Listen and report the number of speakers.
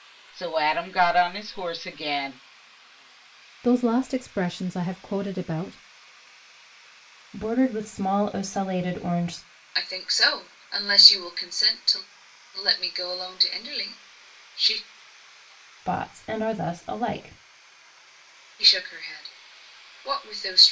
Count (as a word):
four